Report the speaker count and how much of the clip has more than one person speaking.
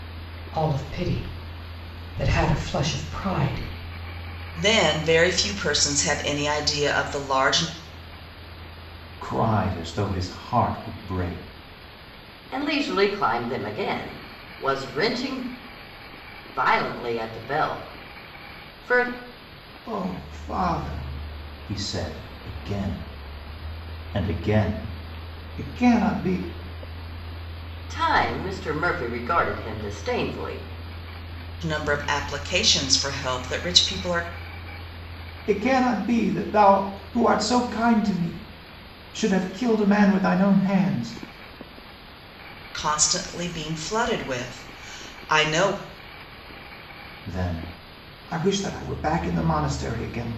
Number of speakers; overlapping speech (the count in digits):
4, no overlap